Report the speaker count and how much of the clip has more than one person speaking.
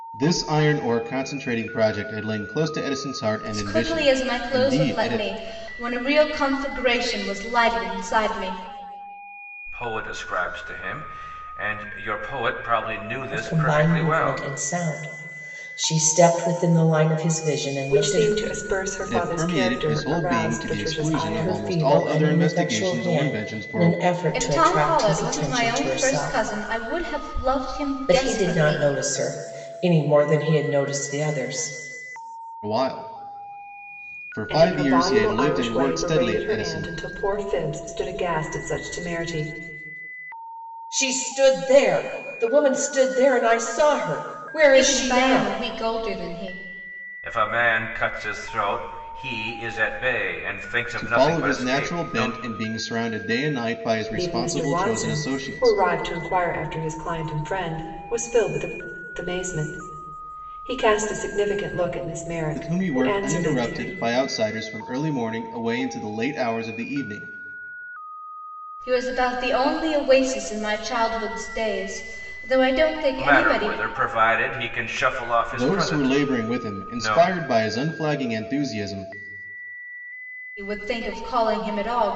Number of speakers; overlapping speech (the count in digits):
5, about 26%